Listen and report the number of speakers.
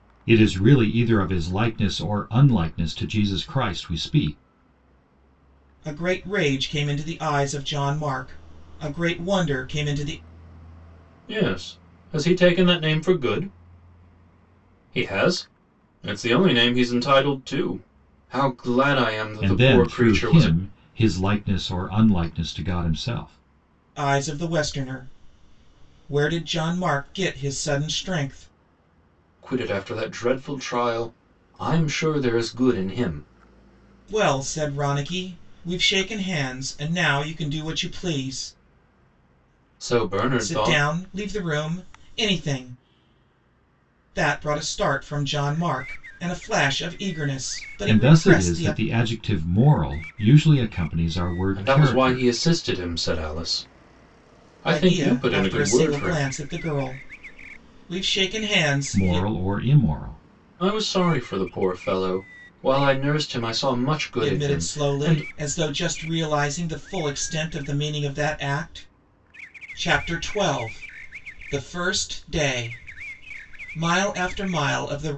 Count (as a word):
three